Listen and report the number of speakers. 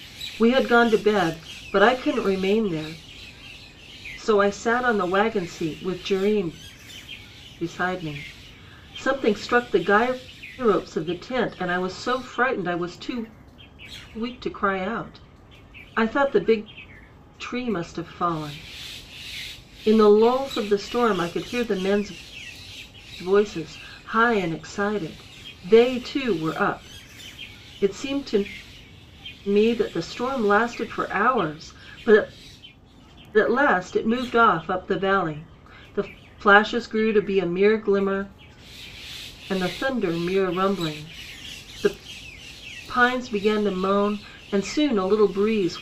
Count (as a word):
one